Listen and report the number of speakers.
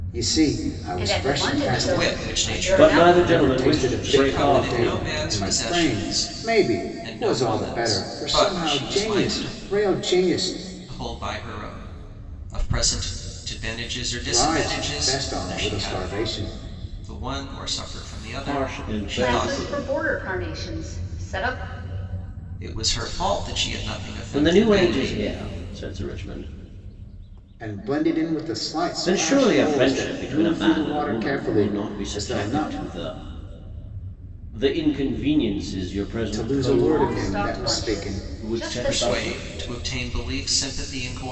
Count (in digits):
4